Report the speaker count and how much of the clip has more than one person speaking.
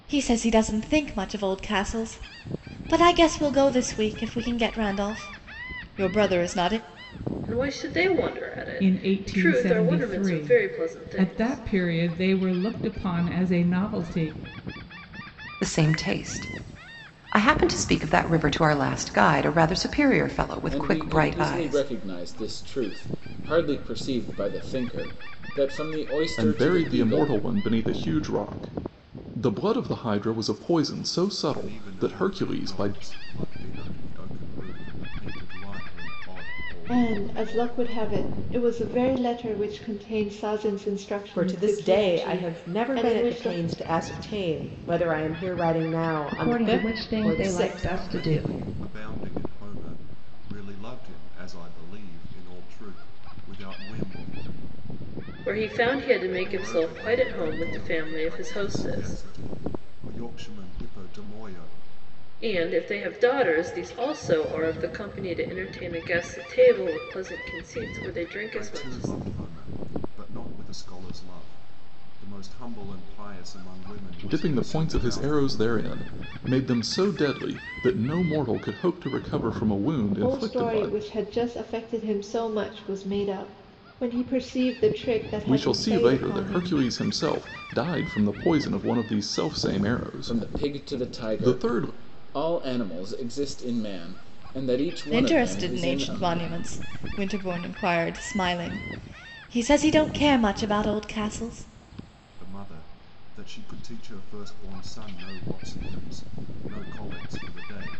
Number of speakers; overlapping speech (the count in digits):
10, about 20%